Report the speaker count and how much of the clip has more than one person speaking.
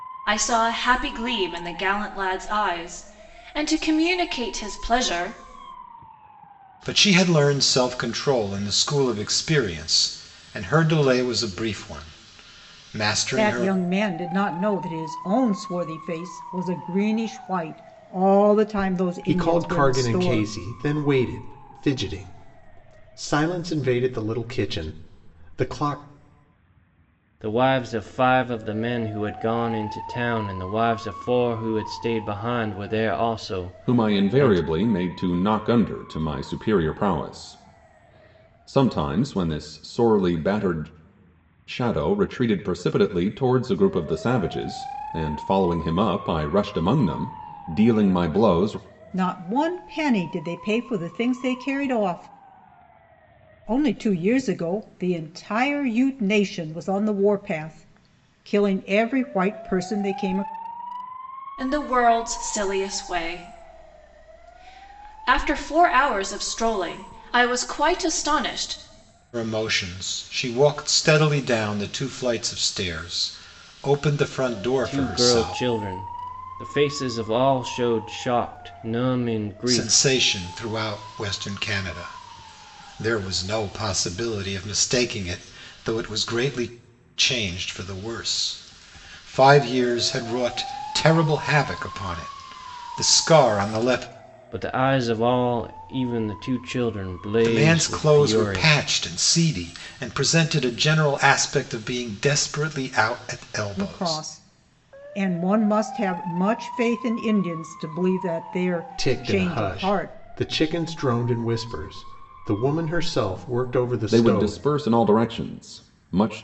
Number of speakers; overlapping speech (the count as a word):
six, about 6%